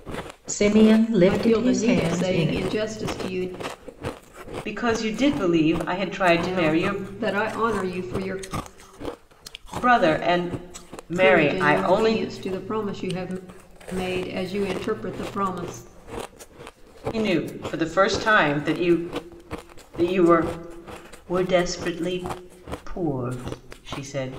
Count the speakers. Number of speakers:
three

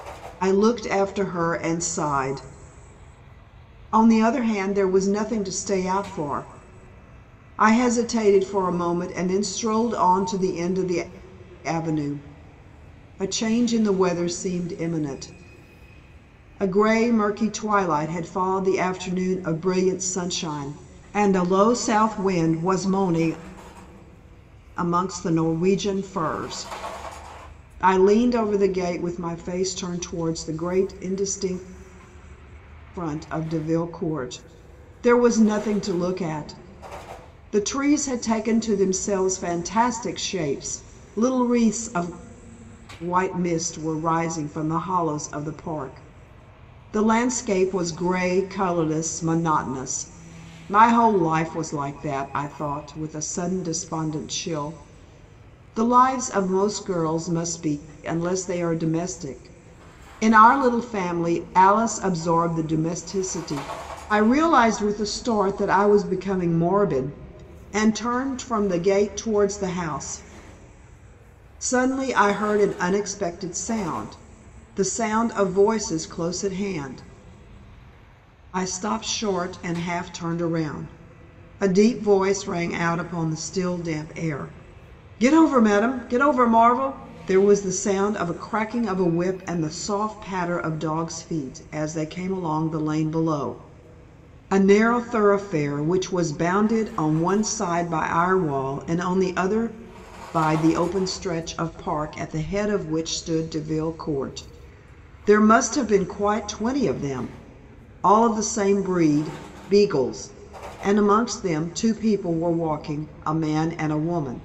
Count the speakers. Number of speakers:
one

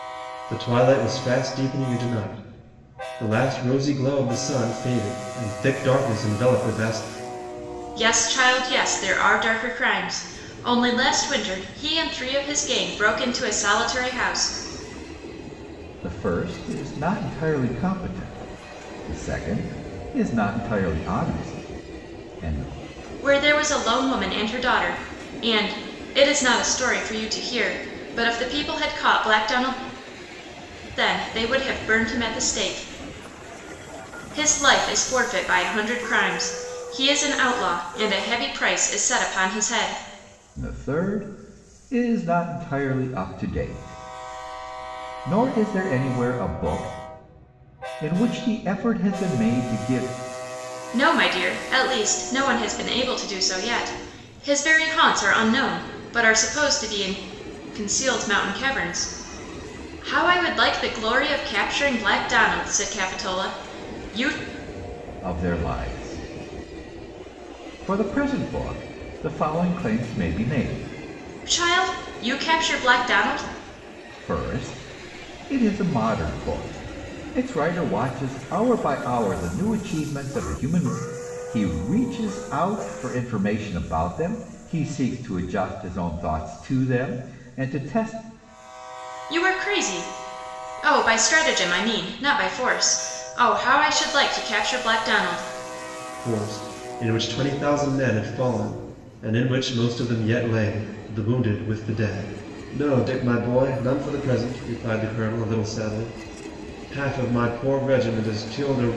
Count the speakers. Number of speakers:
three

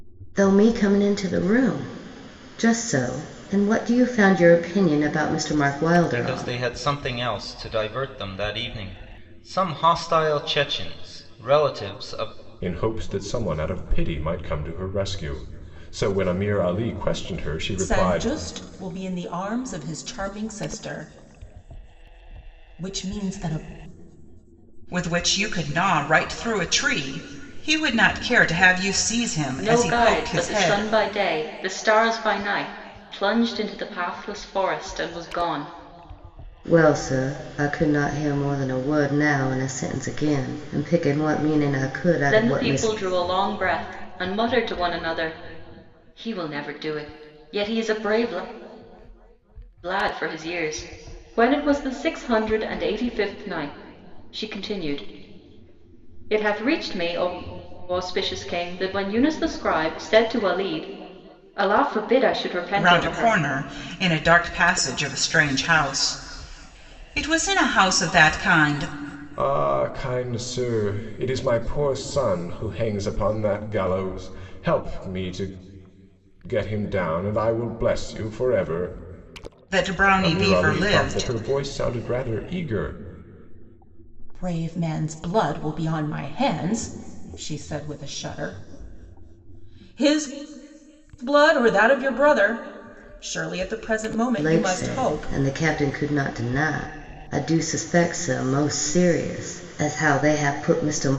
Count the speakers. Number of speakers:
six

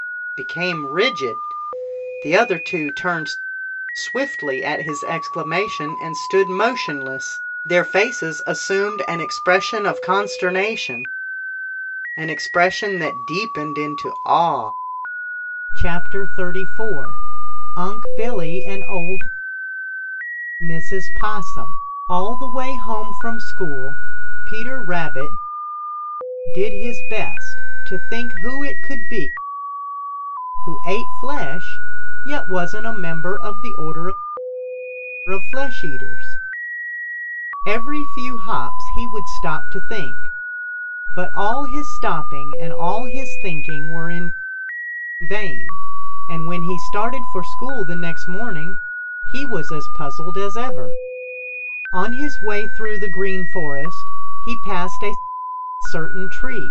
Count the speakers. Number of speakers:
one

